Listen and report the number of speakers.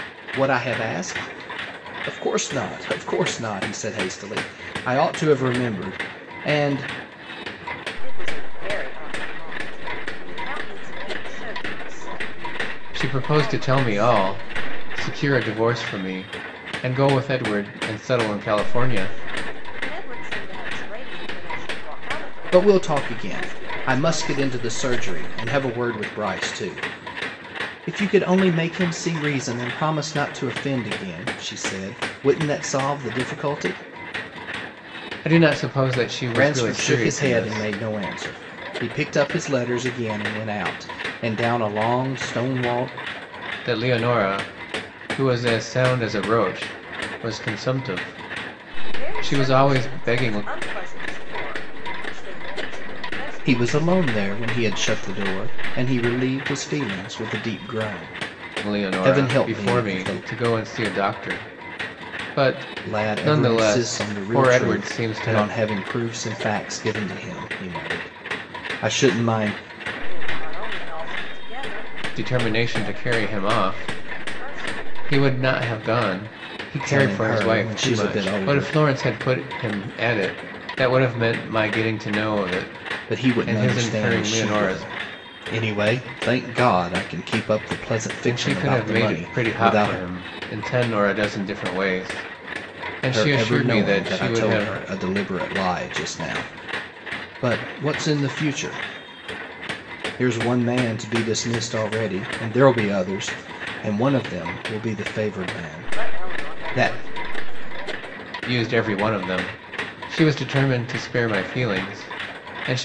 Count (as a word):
three